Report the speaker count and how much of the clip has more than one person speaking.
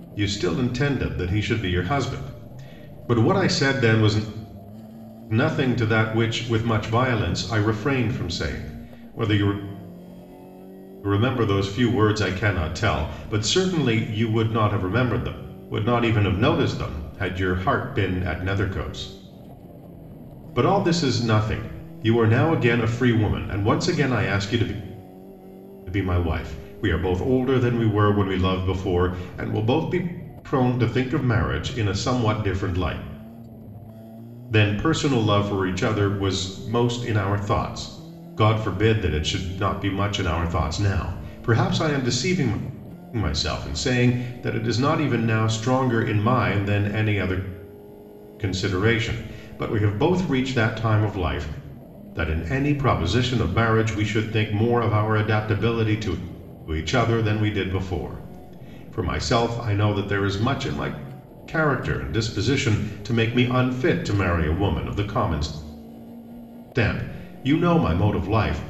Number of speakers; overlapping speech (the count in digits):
1, no overlap